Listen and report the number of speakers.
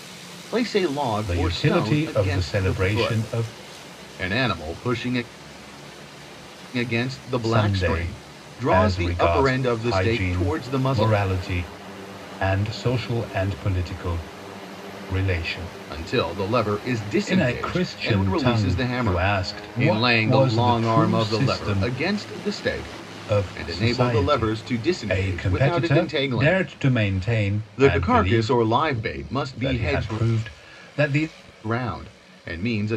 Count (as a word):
two